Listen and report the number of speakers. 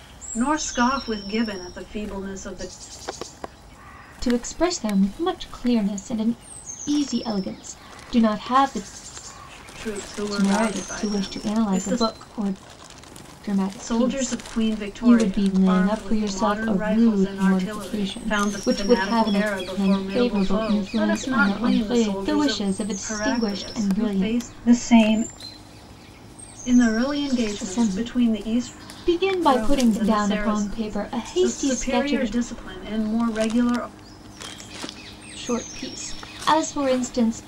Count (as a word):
two